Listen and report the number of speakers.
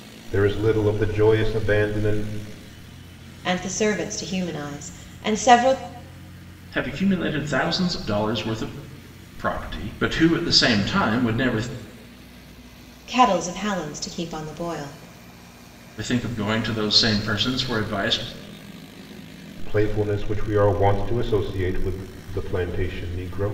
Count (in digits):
3